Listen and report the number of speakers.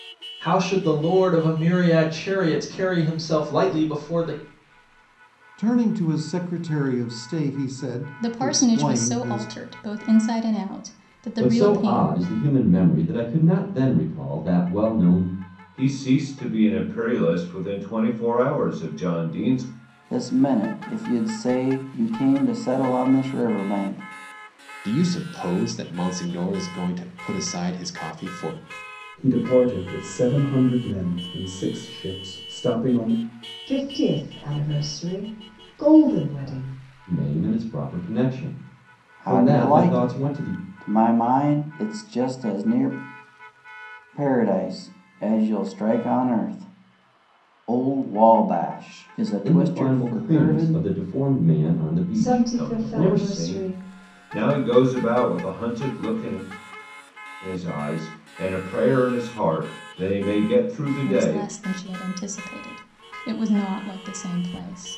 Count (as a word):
nine